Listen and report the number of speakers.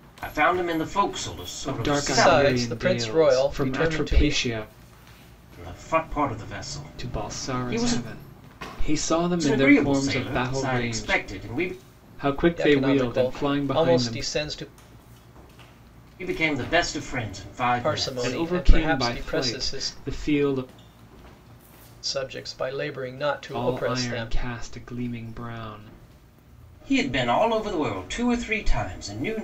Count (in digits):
3